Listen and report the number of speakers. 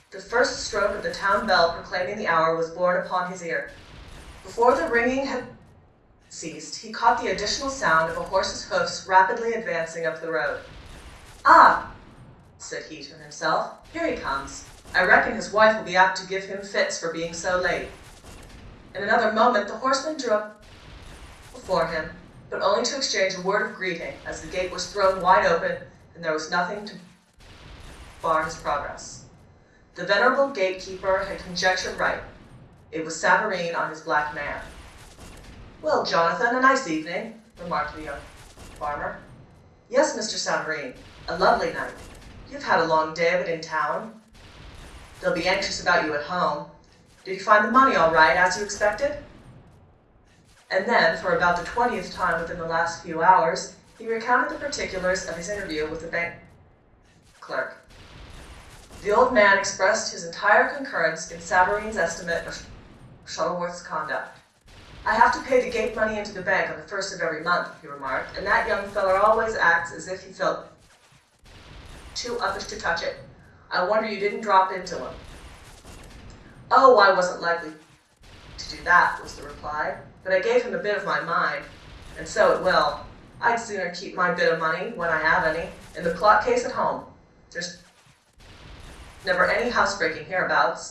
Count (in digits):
1